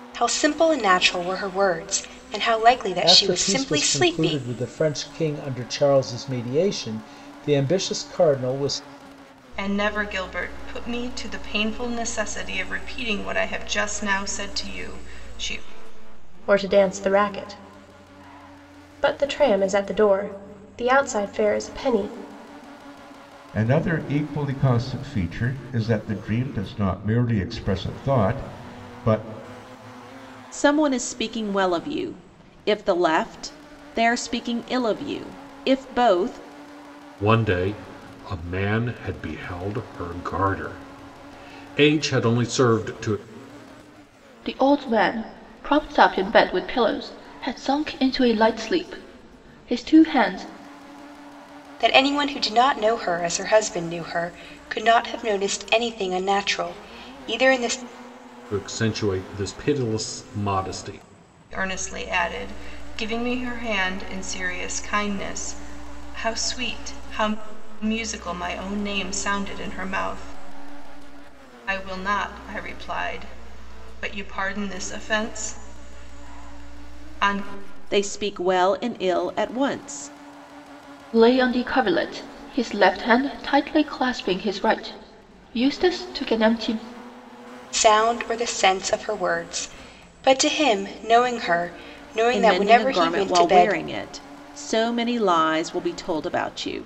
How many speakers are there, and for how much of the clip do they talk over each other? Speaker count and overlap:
8, about 3%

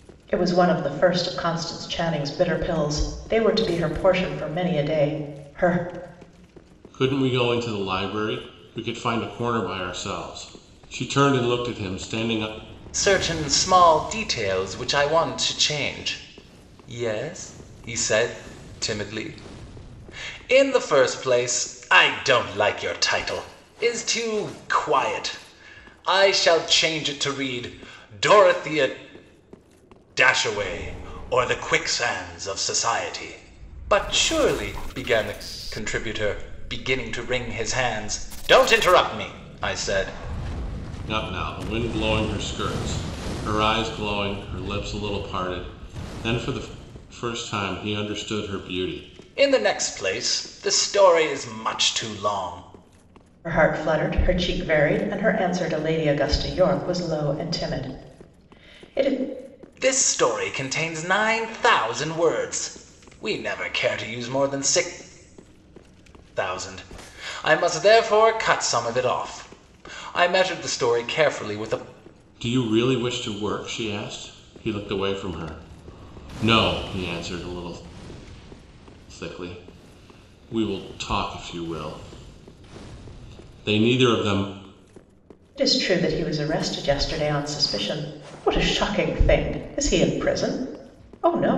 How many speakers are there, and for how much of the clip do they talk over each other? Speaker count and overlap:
3, no overlap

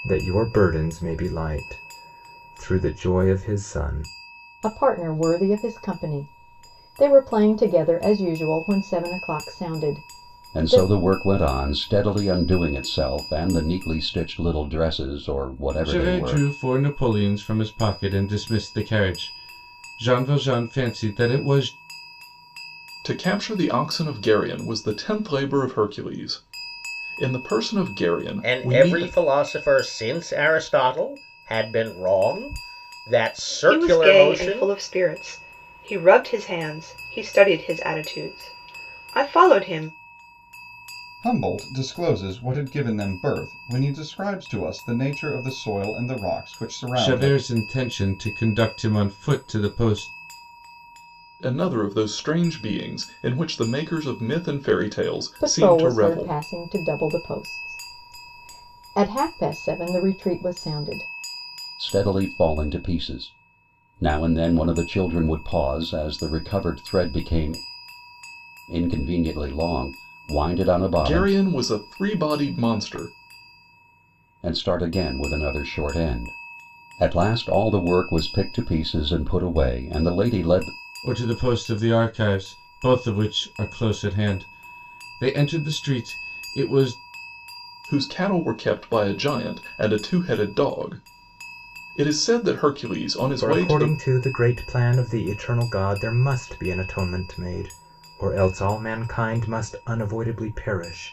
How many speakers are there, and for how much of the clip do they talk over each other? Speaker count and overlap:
8, about 5%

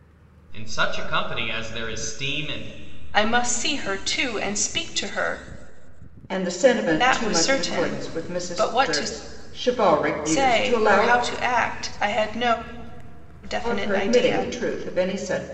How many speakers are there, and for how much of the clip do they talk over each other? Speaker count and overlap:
3, about 25%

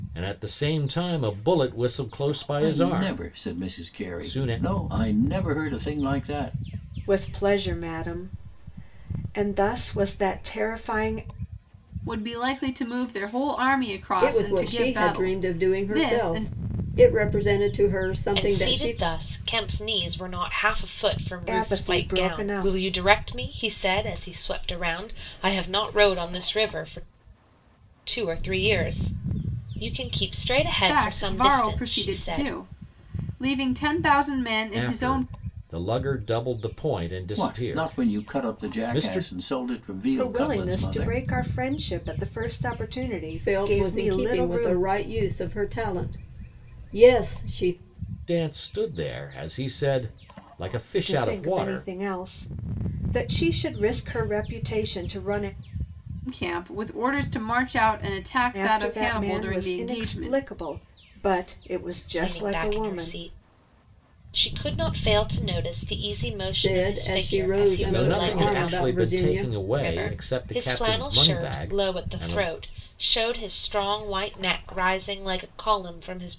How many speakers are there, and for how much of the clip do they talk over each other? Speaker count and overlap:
6, about 30%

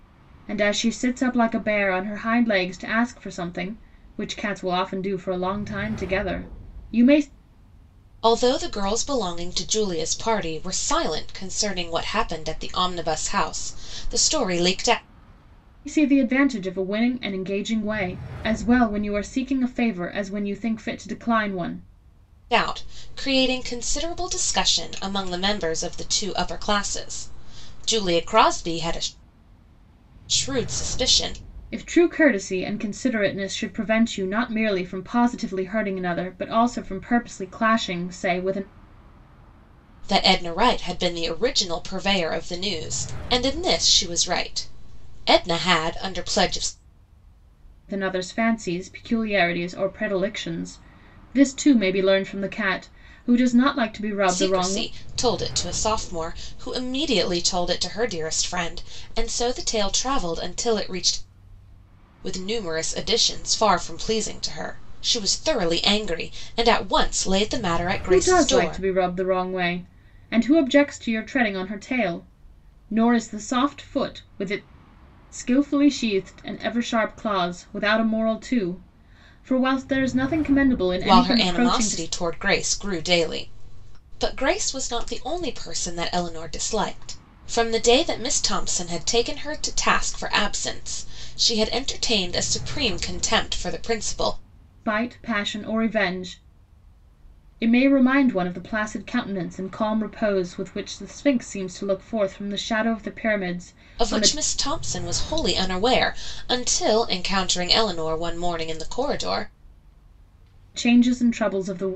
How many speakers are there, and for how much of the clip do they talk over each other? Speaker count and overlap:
2, about 3%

